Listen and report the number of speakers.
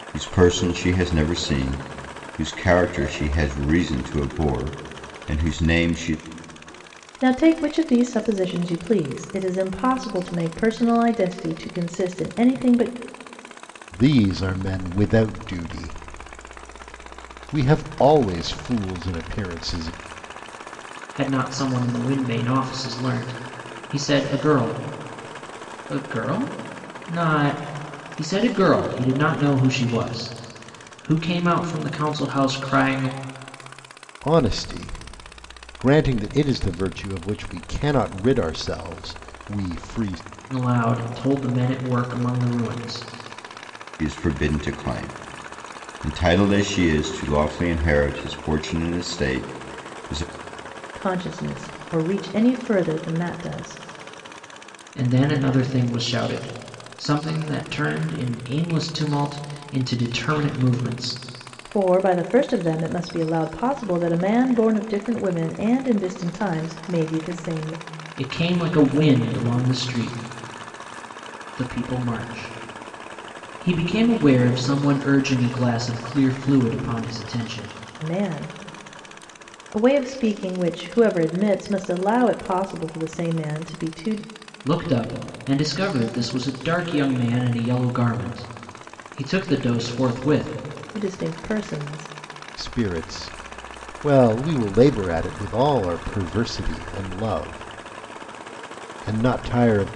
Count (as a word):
four